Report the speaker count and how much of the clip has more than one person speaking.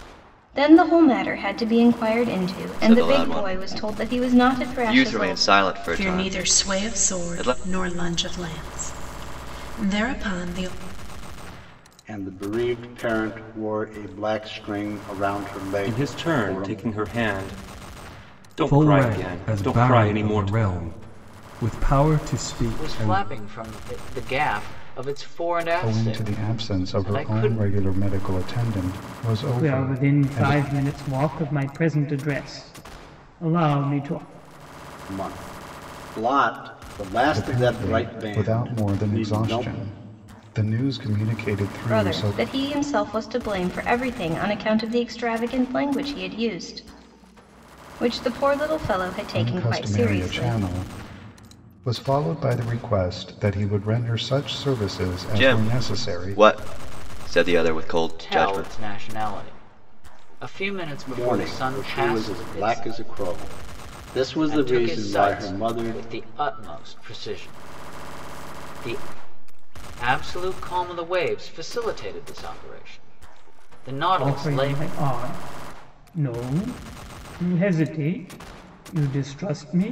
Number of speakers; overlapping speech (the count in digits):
9, about 26%